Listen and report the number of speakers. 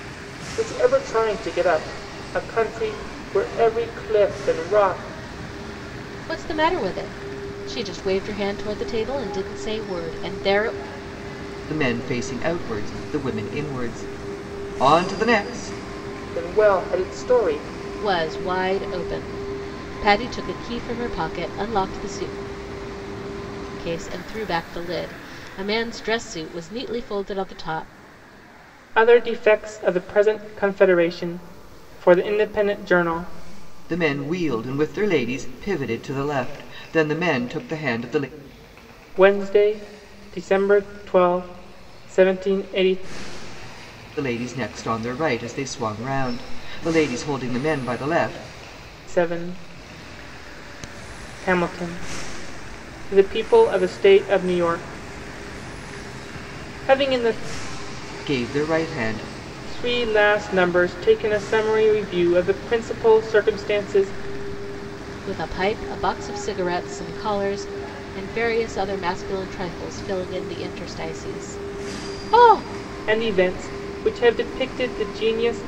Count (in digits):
3